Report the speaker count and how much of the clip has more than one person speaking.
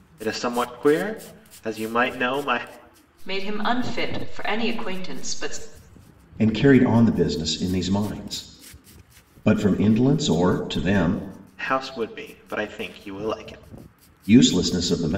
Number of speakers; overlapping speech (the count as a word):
three, no overlap